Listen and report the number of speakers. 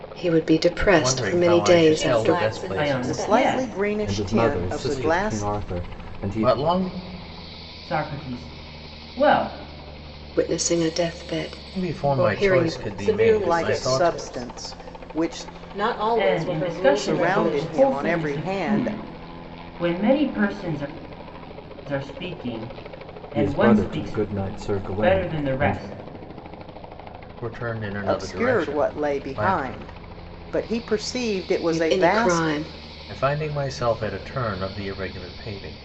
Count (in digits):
6